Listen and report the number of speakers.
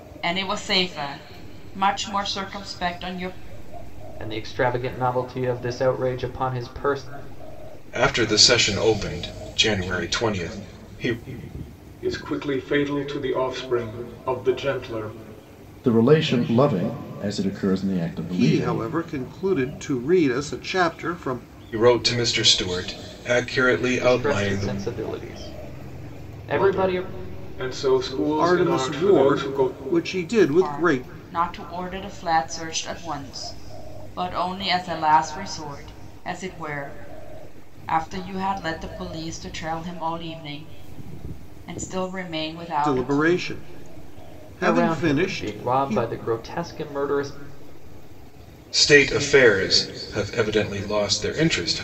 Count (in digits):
6